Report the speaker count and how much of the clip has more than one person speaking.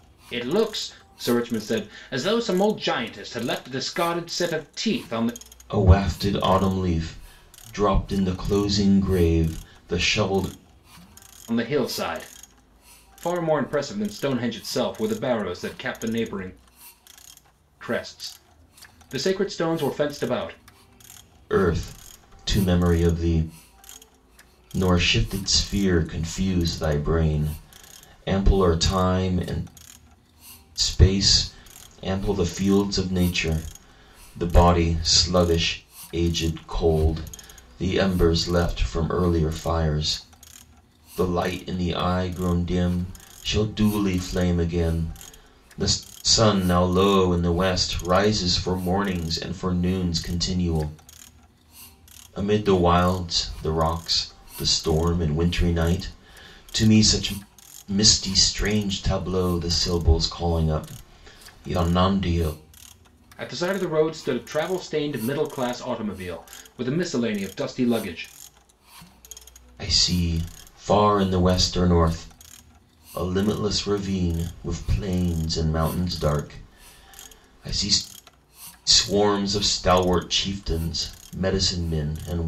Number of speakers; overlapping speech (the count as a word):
two, no overlap